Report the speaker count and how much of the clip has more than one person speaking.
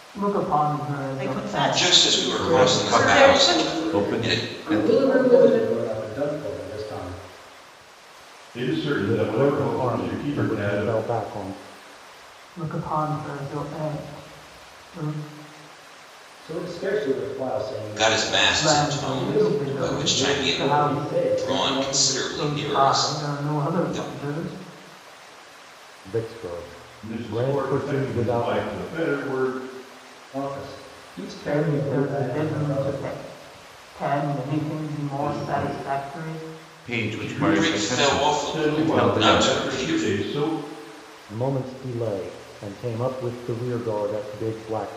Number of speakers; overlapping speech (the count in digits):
8, about 45%